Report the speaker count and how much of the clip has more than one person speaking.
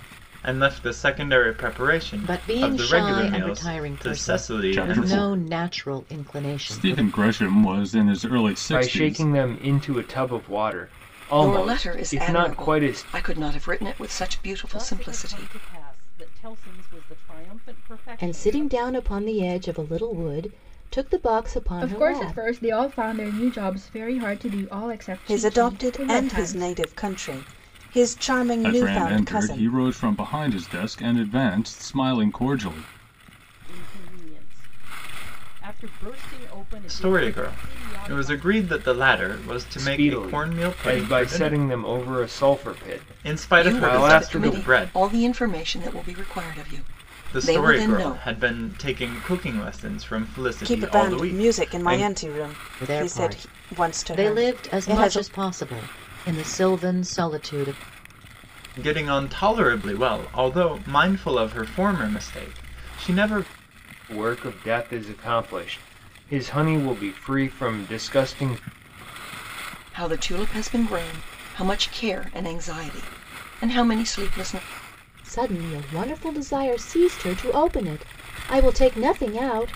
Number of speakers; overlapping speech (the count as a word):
nine, about 28%